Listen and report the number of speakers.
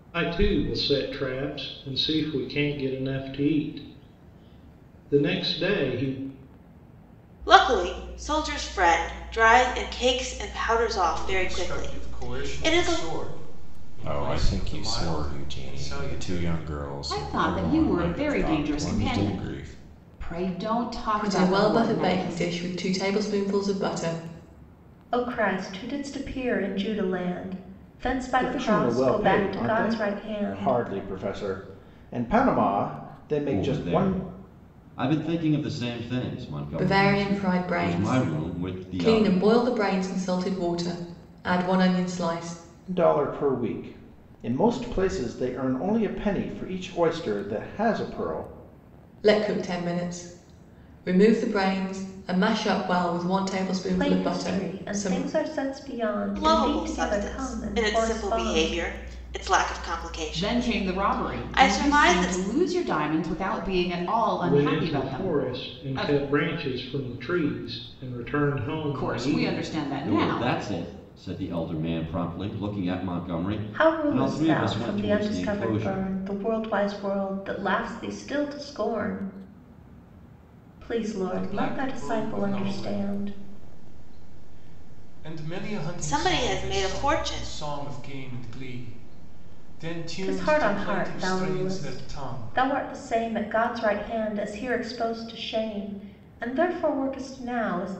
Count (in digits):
9